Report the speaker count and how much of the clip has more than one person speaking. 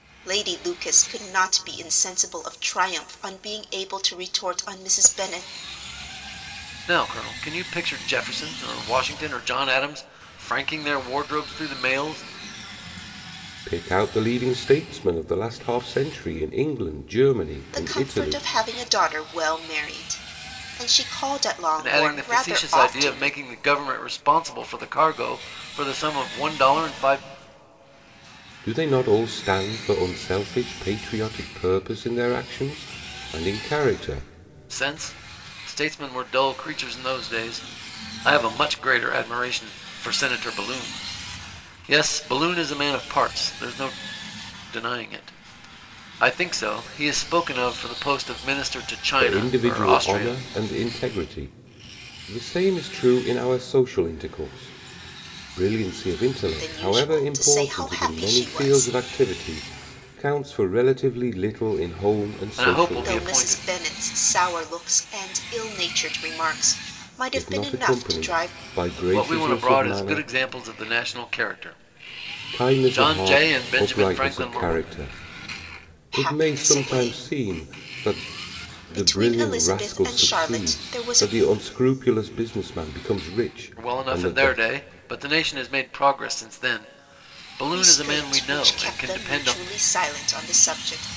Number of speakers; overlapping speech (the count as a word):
three, about 21%